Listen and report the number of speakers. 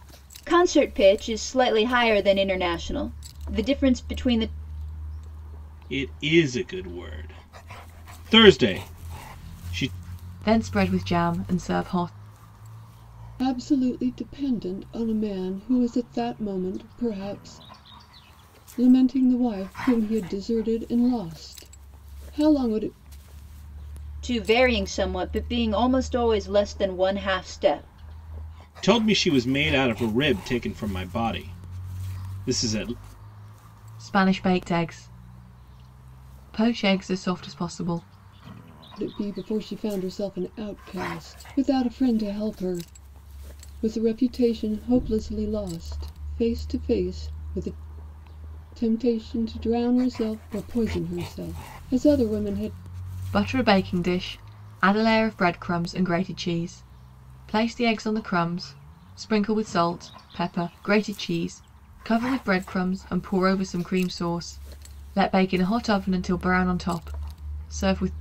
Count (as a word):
four